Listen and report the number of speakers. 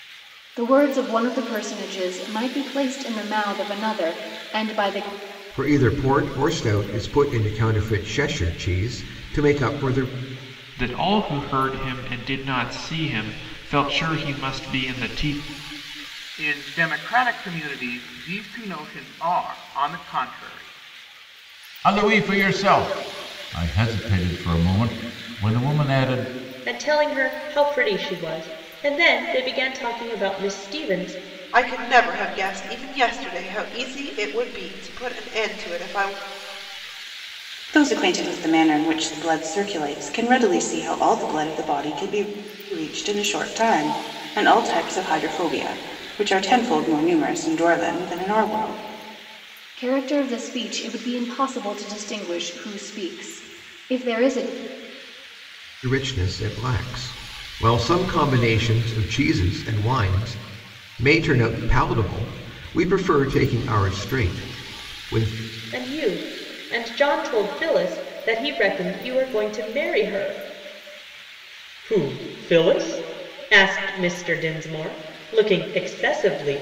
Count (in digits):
8